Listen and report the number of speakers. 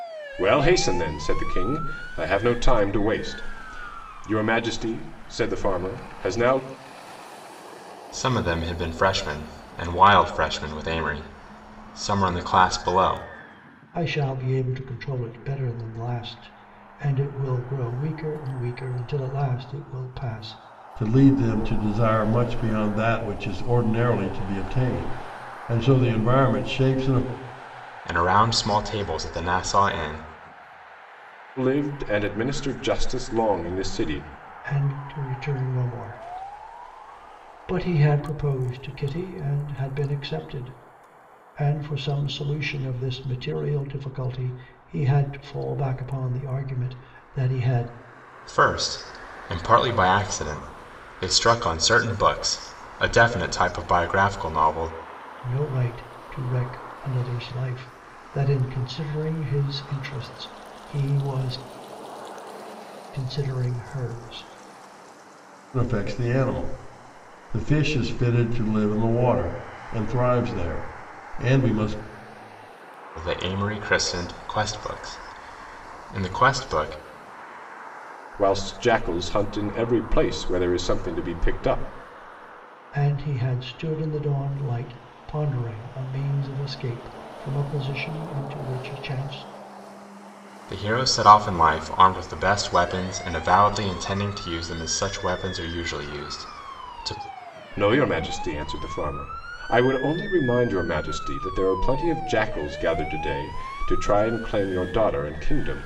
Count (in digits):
4